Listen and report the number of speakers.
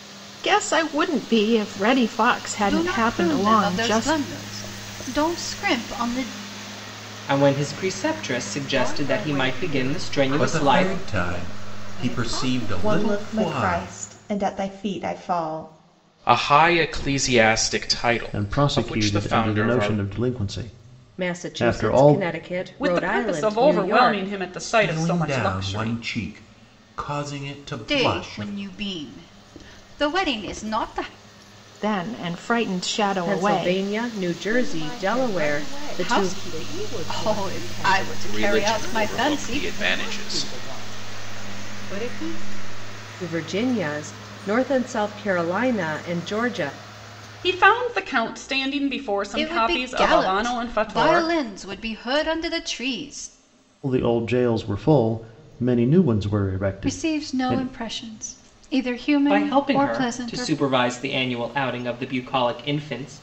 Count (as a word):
ten